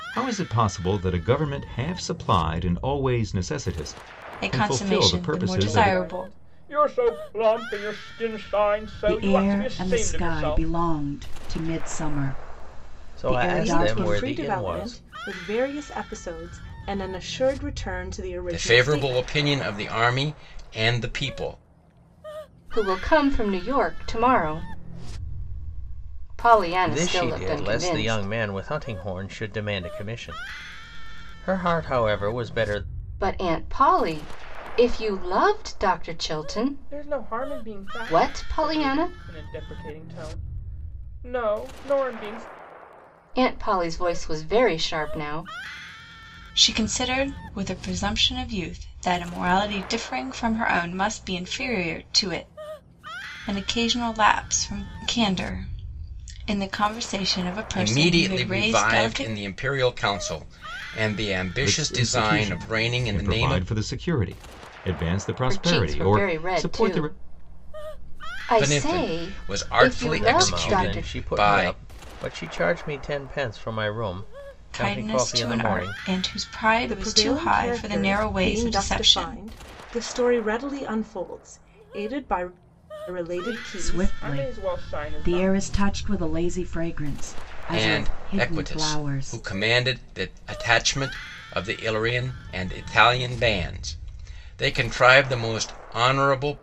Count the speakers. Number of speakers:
eight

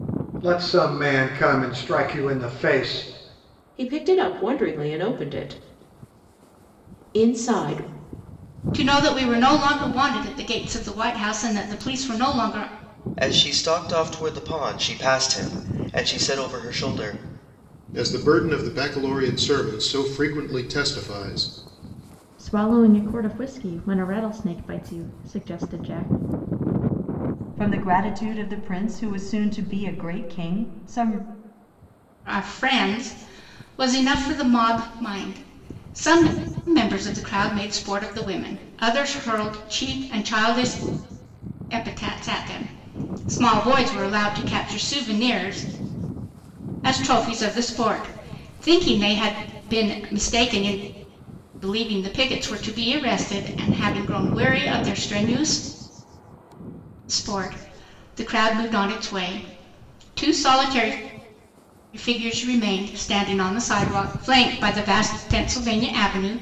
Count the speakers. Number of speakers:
seven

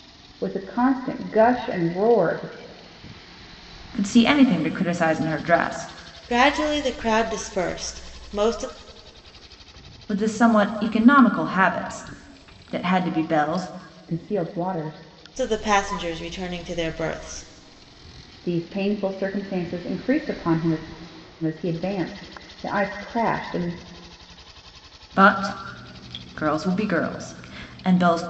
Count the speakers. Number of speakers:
three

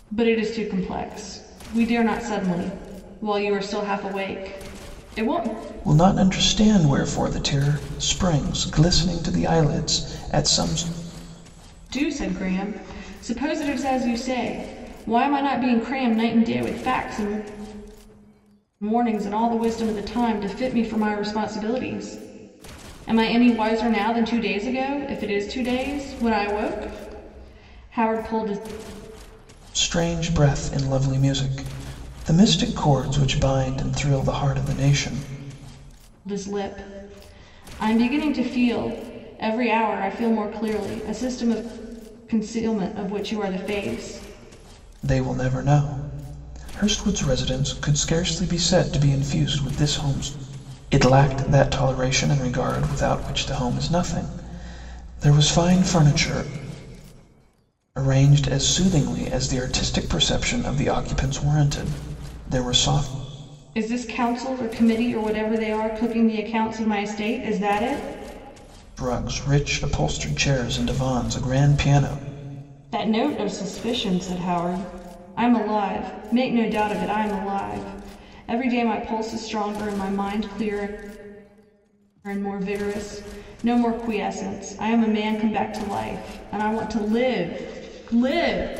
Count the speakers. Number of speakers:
two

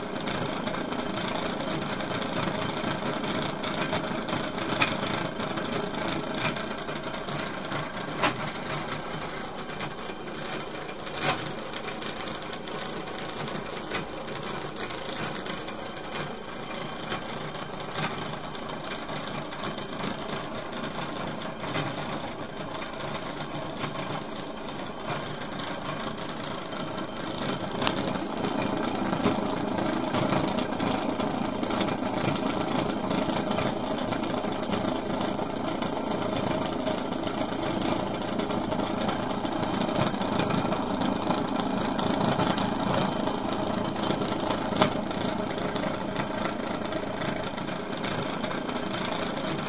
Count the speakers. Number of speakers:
zero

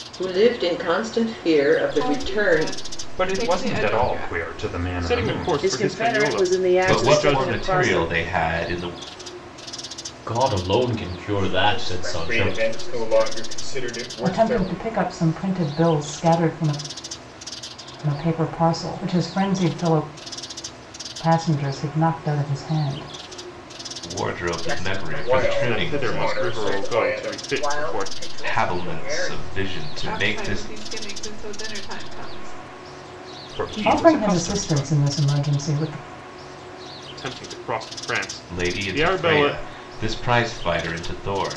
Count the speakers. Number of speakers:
ten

